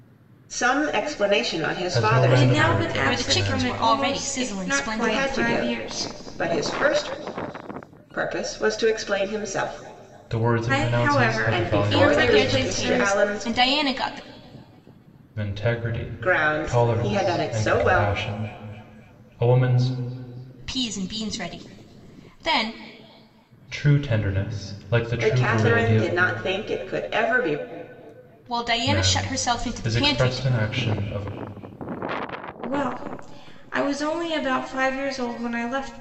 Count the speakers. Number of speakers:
4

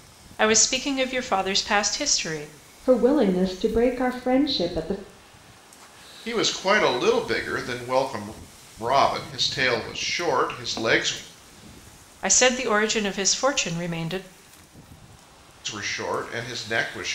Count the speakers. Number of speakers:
3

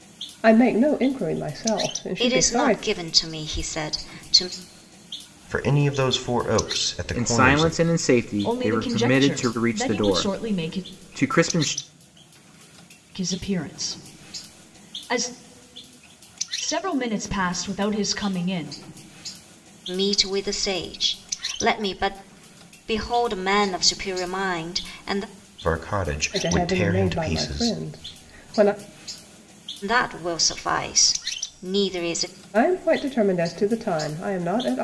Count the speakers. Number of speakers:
5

